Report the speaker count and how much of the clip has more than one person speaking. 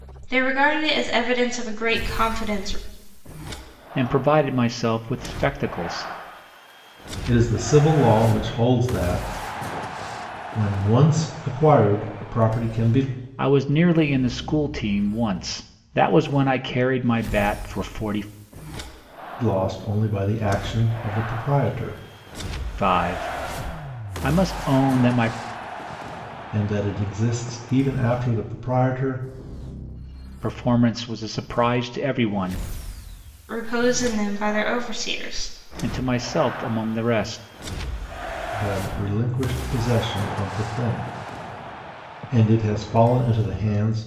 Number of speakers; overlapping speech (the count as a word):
three, no overlap